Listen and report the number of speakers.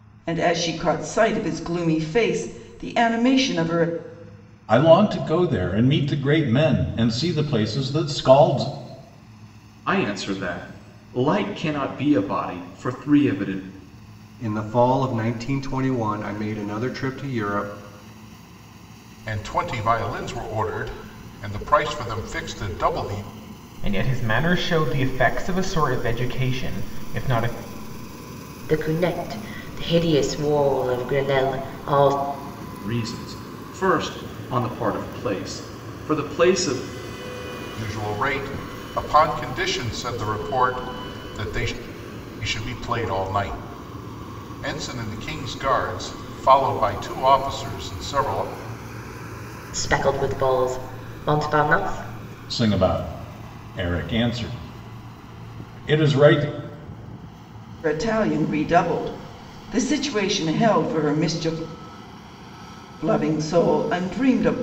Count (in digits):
7